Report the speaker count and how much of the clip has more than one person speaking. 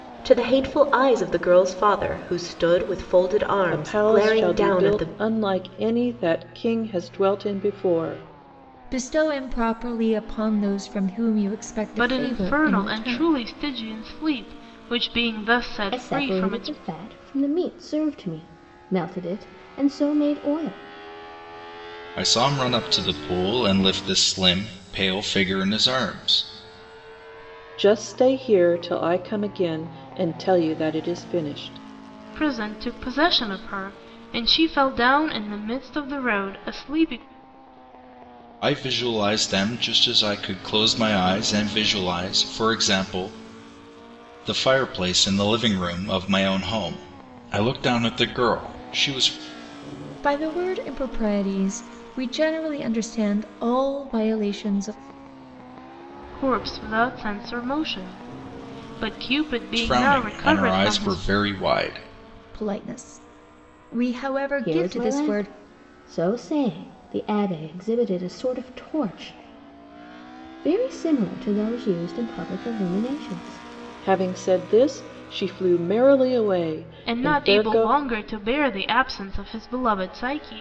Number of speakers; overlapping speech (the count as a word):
six, about 9%